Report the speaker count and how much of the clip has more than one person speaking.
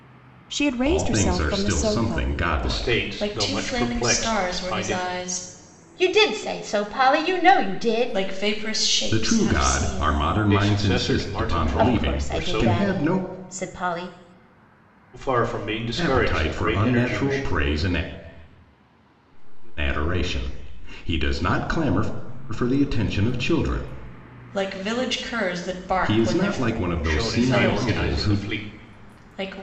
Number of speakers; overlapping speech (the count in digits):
6, about 56%